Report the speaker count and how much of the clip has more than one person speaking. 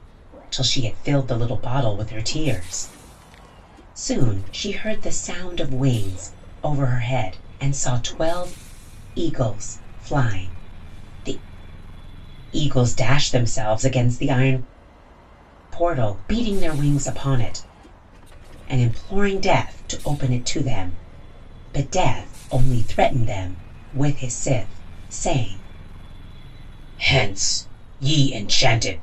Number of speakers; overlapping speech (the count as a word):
one, no overlap